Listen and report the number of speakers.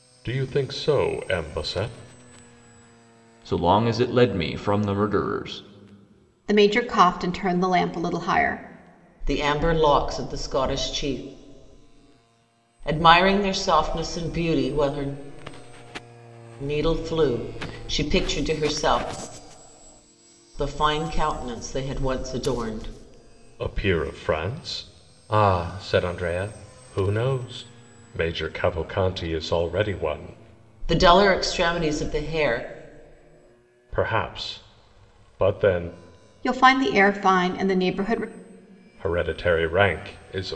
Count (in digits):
4